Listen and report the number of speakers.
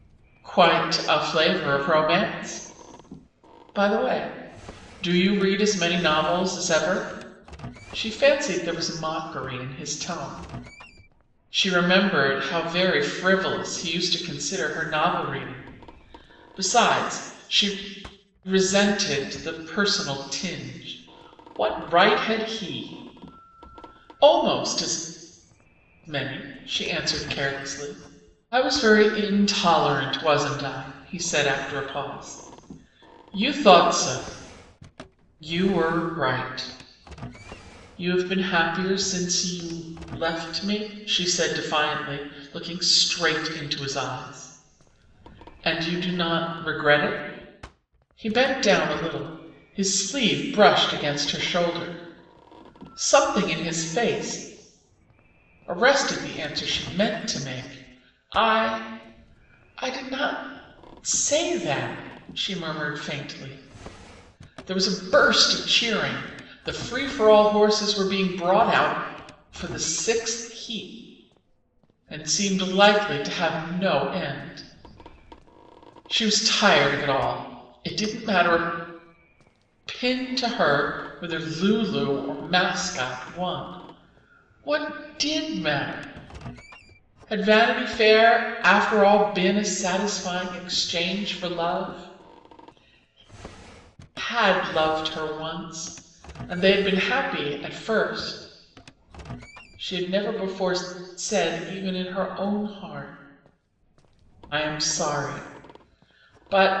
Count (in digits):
1